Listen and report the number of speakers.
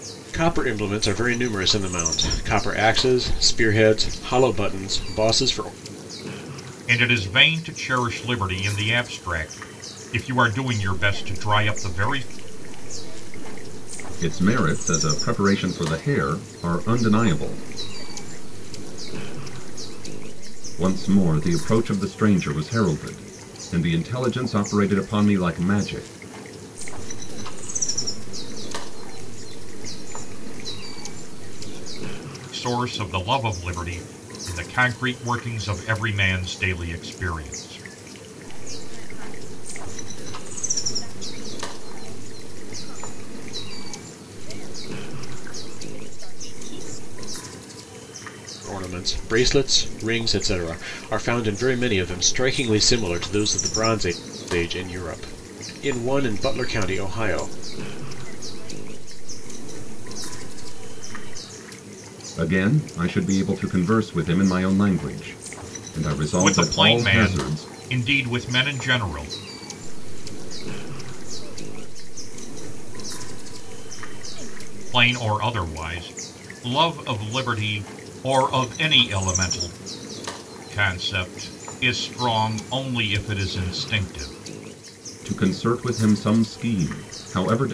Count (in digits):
4